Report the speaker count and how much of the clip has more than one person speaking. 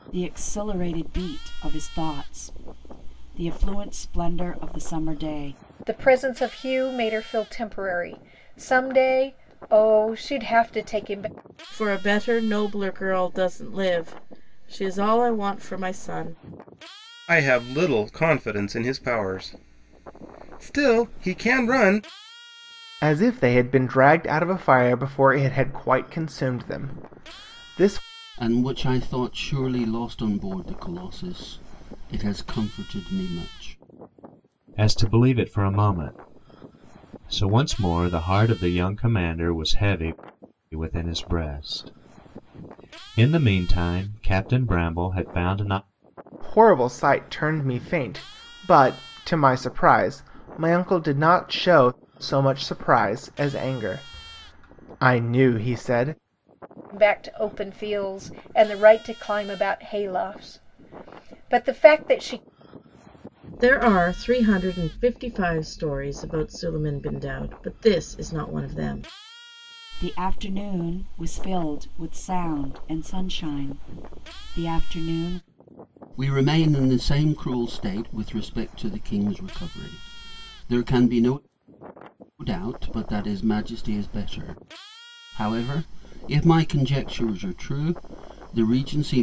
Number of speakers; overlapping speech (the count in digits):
7, no overlap